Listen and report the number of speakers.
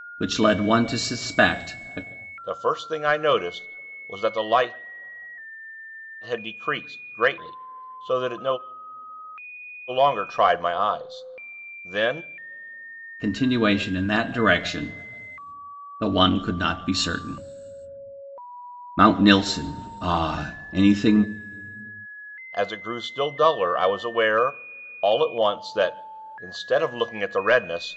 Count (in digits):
2